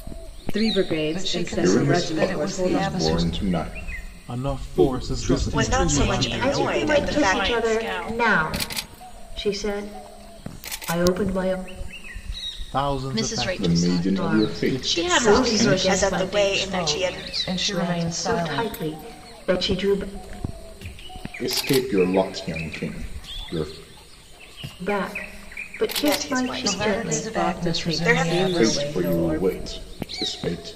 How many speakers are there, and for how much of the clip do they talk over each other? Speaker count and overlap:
8, about 49%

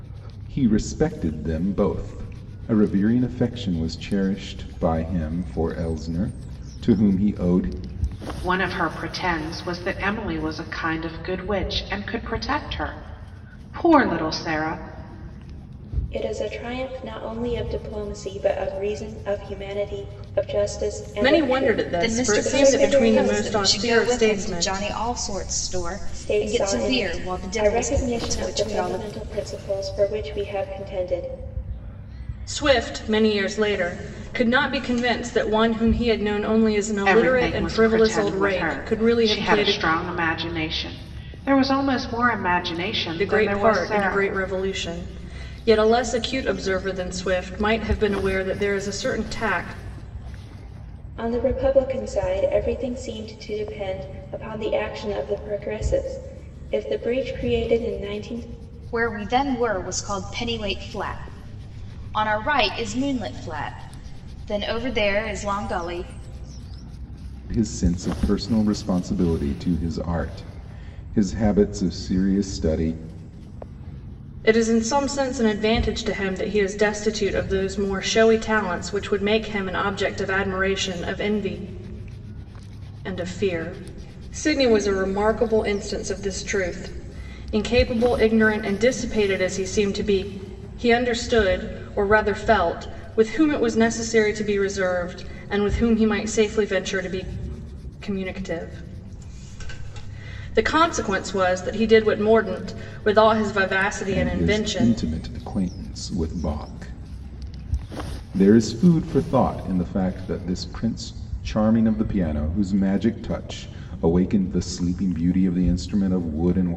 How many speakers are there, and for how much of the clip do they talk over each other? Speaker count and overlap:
5, about 10%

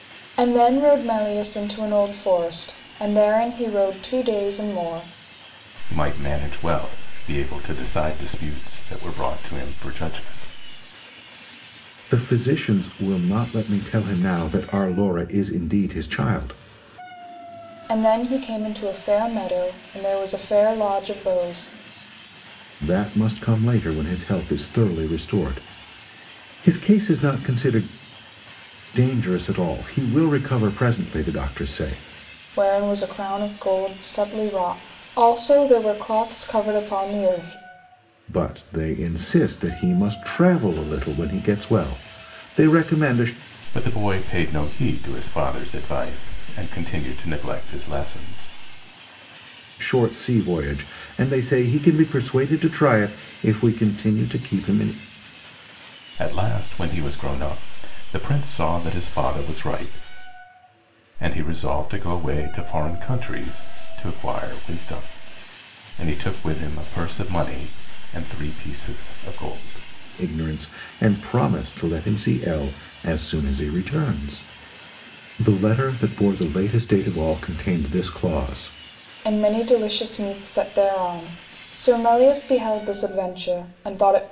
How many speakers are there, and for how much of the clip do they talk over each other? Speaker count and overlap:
3, no overlap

